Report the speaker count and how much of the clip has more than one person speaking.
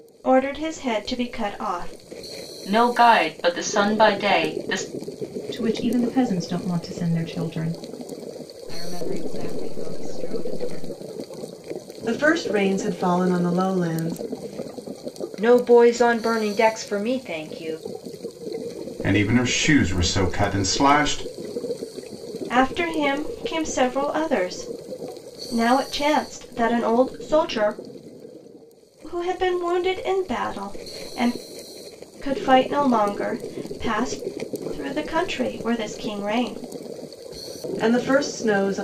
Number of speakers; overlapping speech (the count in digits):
7, no overlap